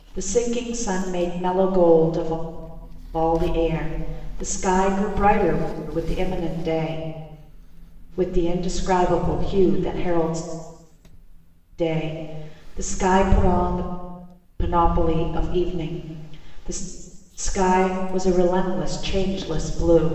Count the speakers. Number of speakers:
1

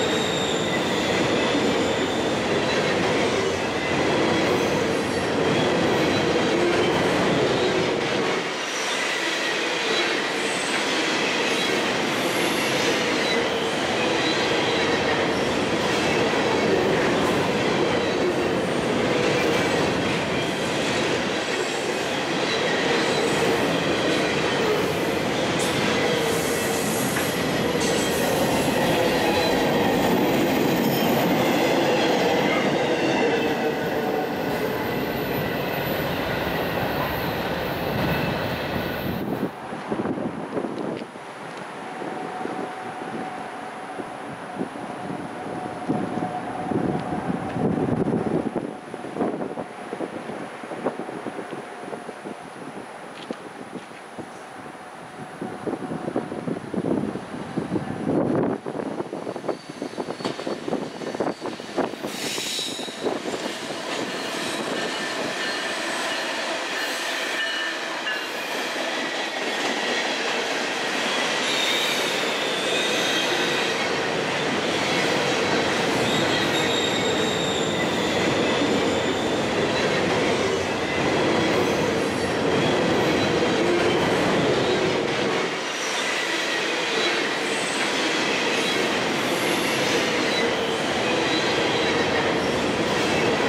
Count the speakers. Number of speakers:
0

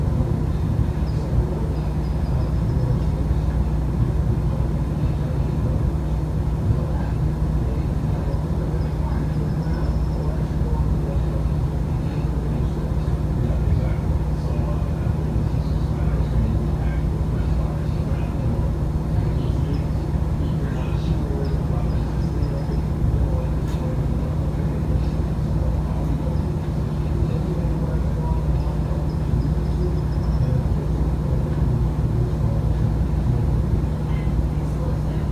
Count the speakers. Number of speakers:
0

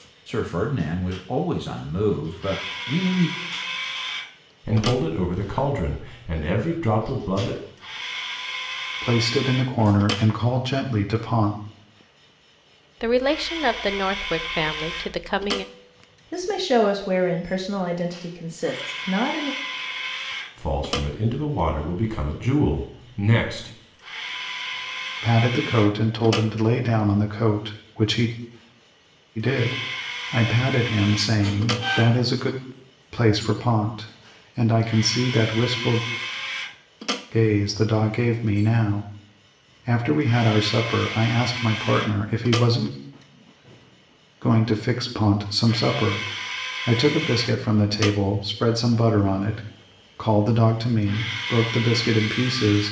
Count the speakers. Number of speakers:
5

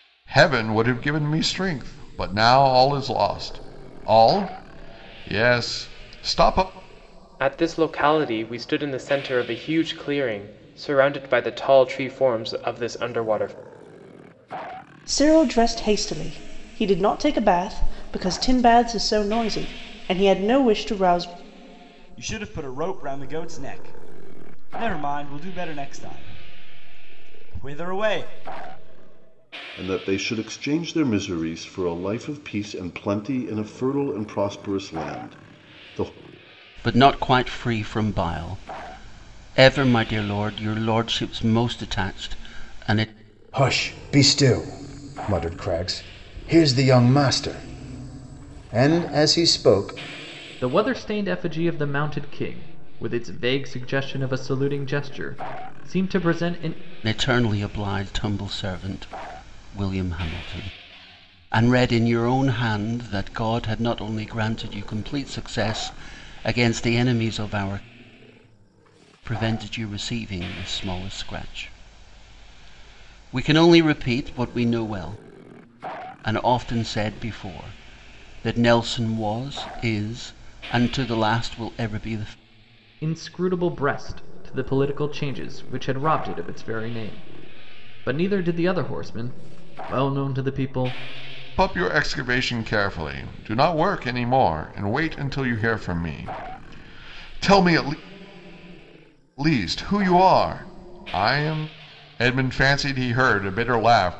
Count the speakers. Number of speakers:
8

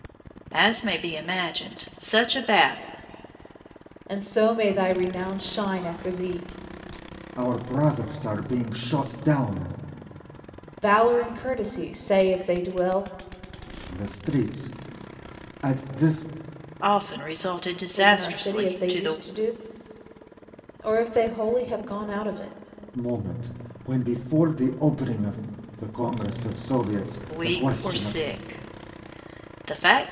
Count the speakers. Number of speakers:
3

